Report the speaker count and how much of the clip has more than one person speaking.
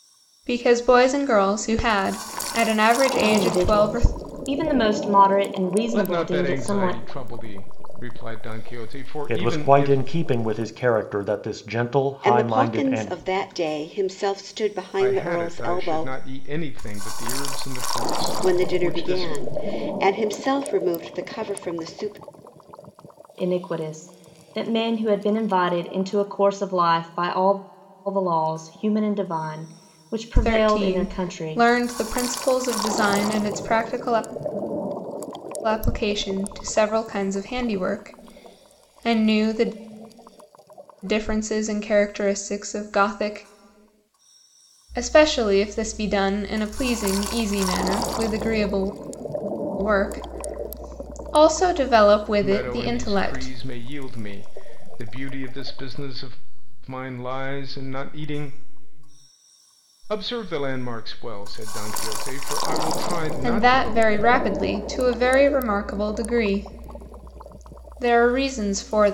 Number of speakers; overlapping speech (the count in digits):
5, about 13%